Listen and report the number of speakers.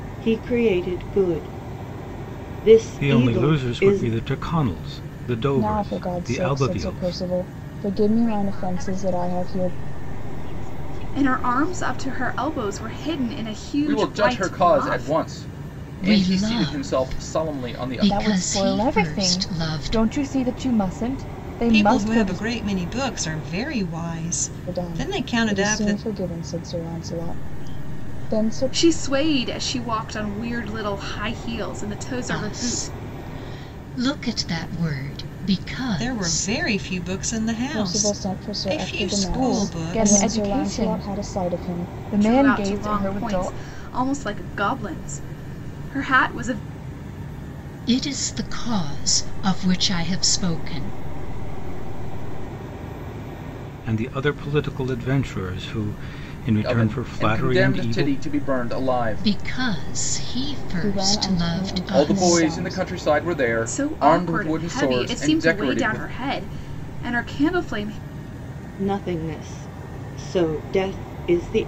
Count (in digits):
9